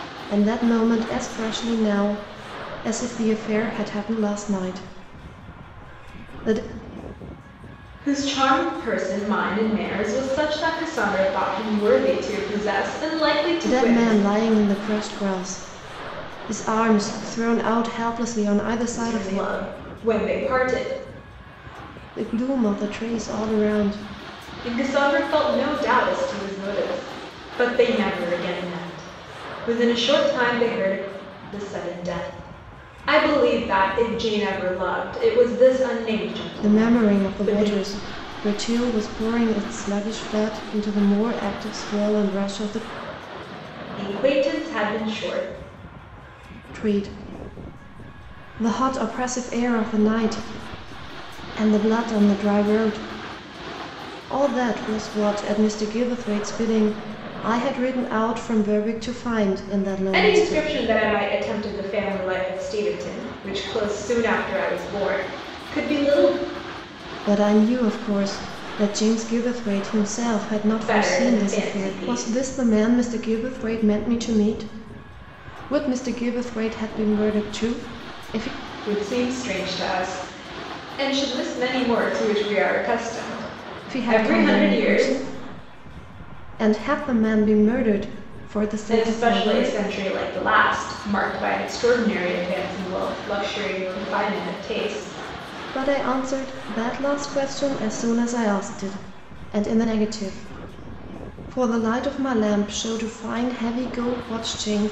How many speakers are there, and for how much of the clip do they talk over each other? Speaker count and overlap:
2, about 7%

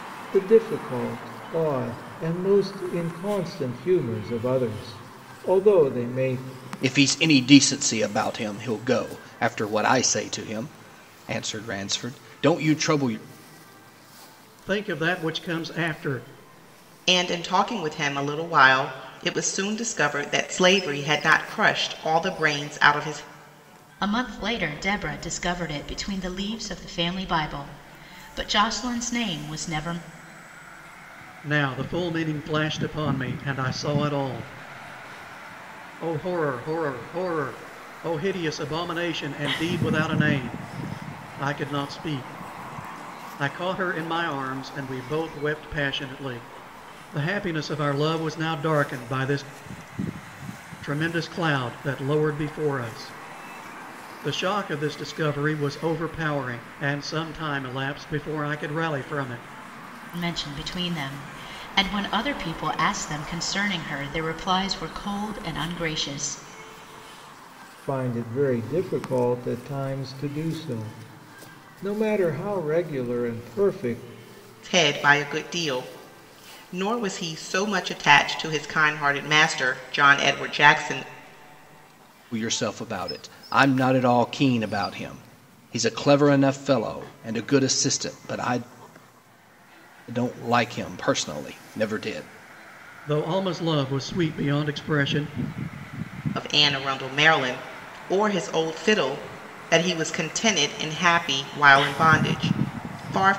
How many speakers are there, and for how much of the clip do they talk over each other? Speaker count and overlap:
5, no overlap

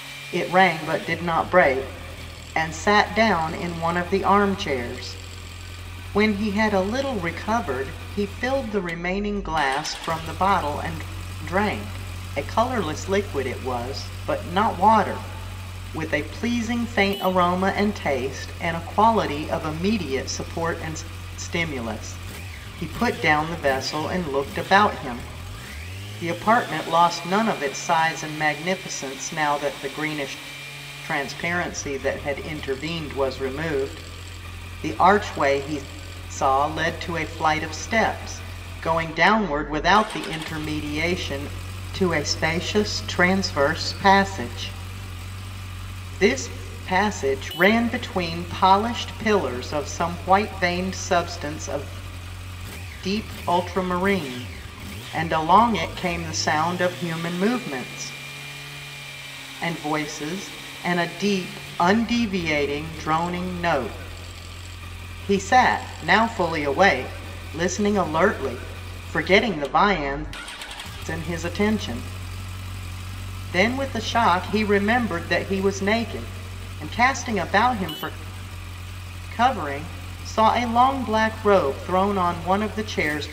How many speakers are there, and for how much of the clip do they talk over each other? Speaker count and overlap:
1, no overlap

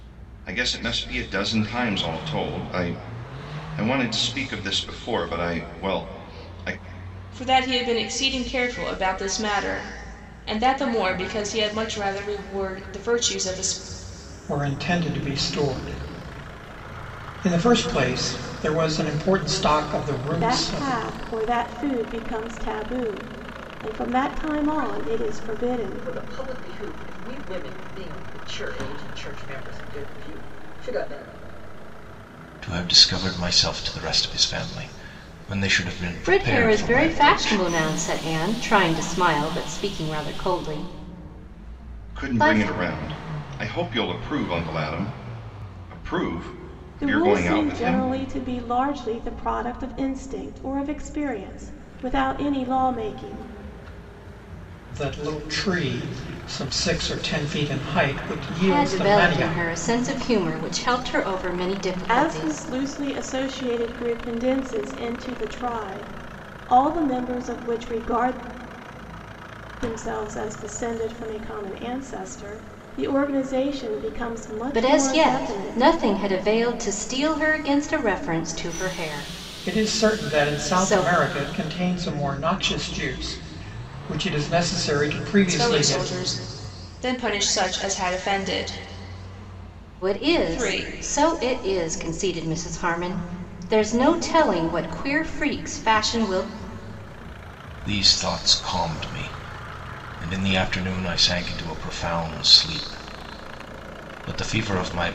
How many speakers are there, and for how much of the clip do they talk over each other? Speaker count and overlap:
7, about 11%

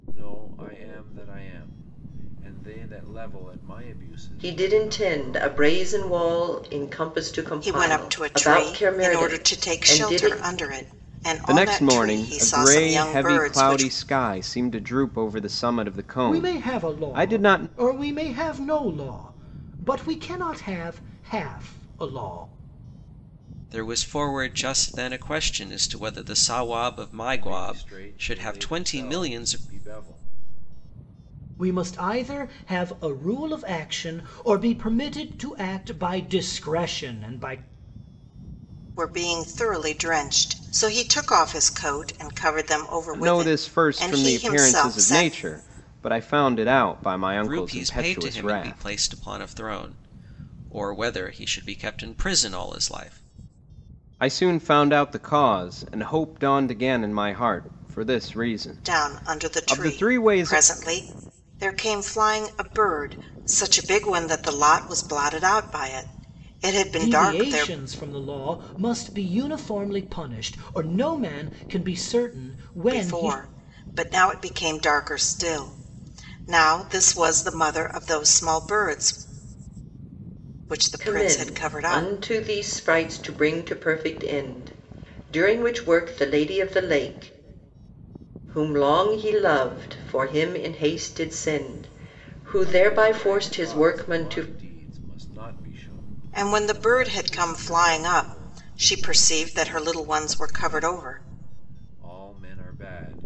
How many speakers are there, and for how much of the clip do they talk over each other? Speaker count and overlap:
6, about 23%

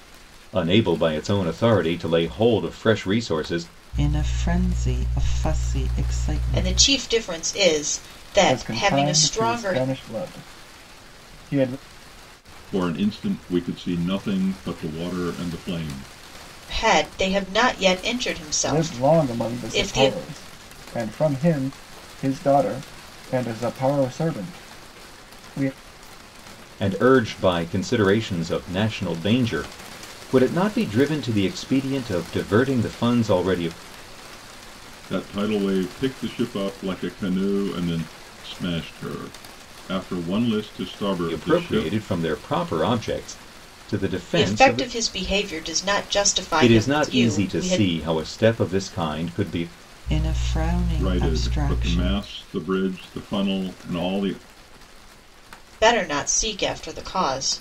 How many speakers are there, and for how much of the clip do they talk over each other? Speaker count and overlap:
5, about 12%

